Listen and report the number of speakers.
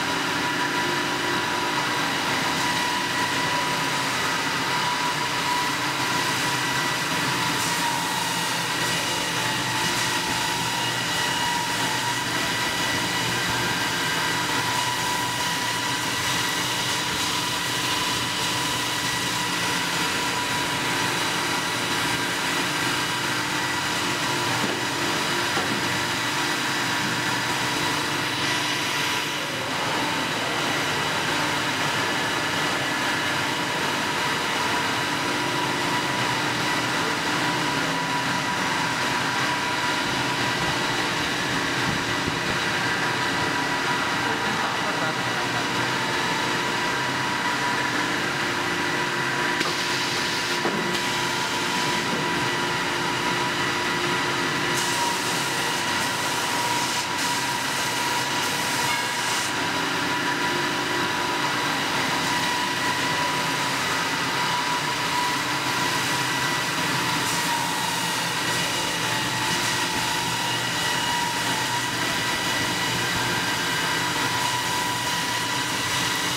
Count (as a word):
zero